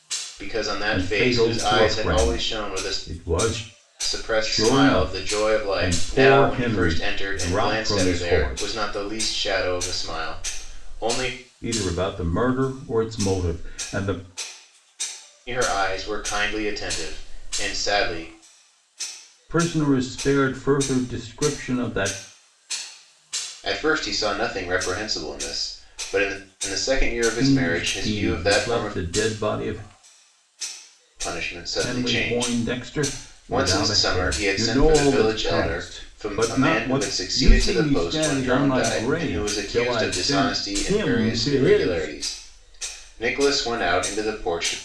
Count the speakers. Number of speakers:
two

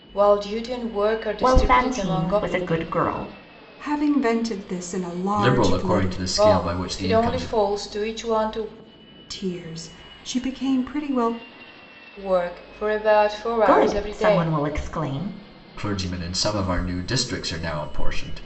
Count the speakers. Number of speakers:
four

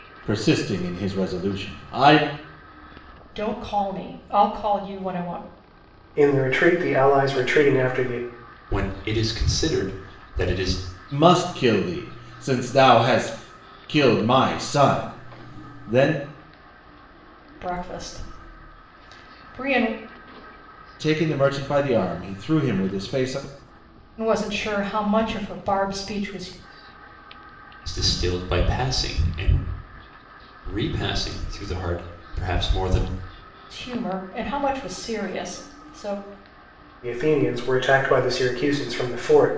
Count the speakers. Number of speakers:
four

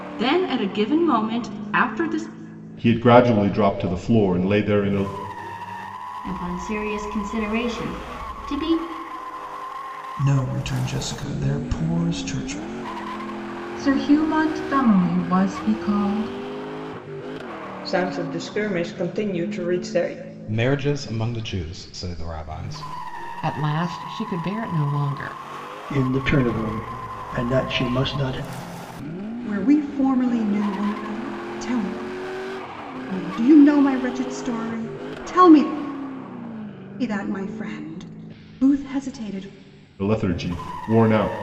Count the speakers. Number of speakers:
ten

